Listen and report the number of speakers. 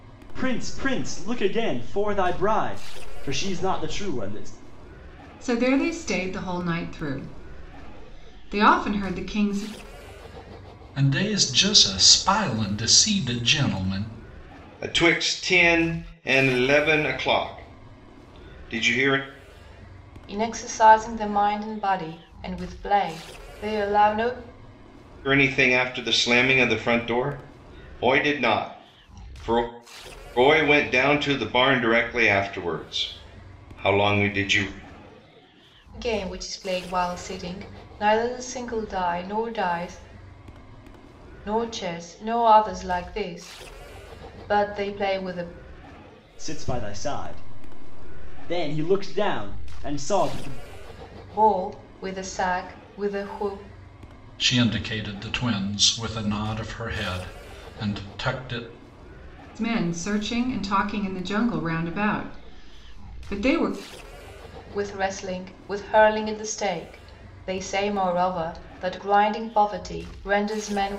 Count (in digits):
5